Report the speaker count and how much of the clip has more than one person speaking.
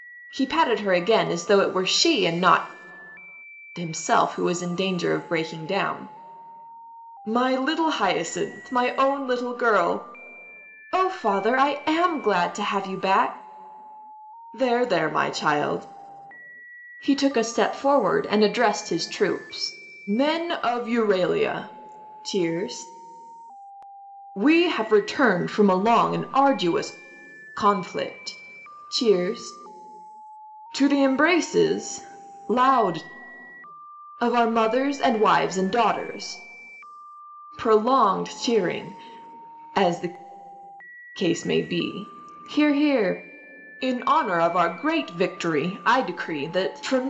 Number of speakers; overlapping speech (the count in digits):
1, no overlap